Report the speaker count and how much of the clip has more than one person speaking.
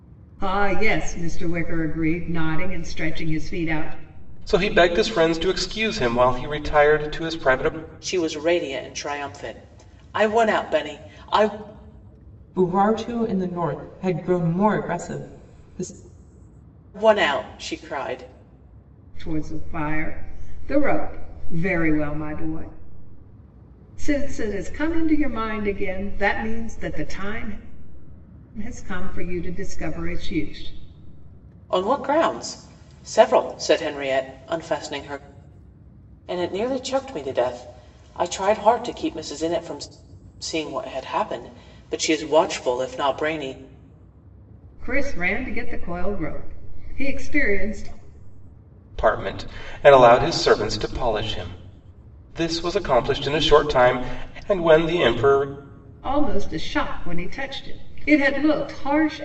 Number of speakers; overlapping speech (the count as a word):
four, no overlap